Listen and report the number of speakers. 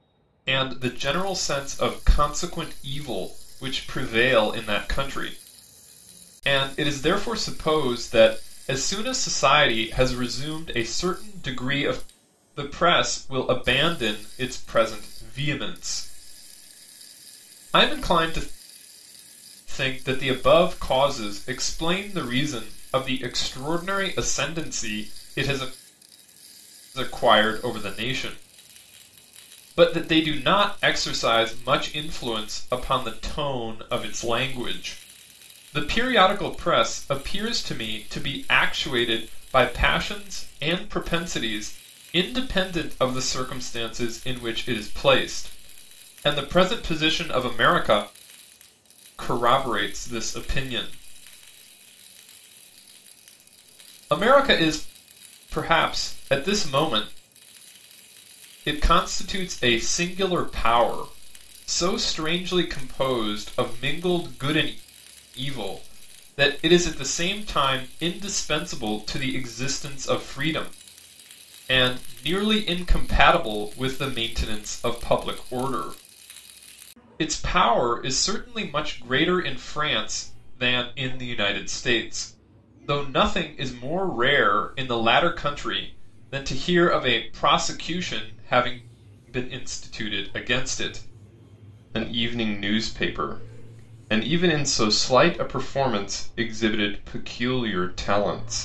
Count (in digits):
1